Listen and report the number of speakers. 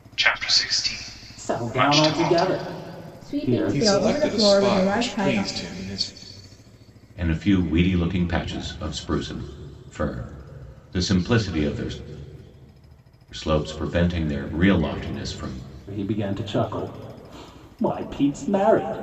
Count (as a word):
five